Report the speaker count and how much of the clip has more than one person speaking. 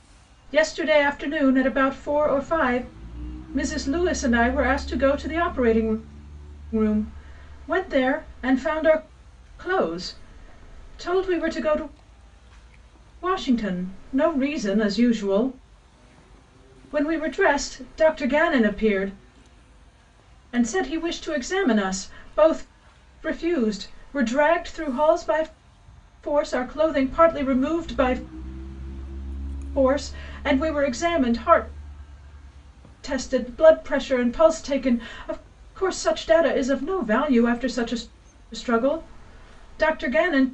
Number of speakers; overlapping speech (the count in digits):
1, no overlap